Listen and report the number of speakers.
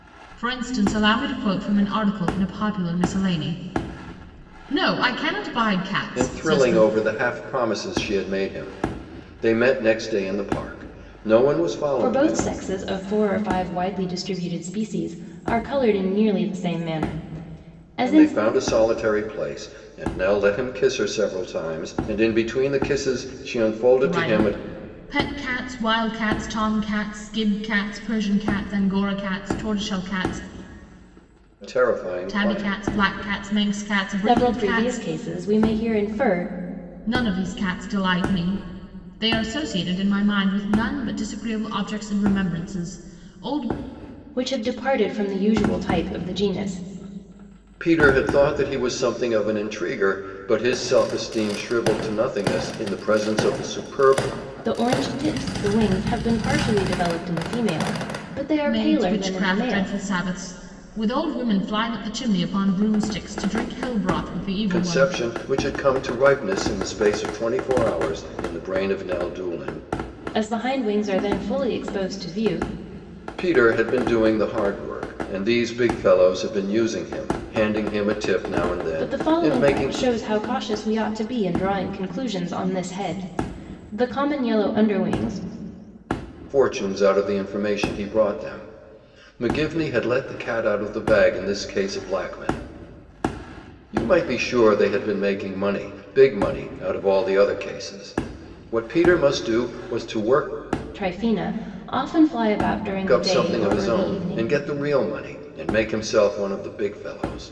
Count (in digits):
3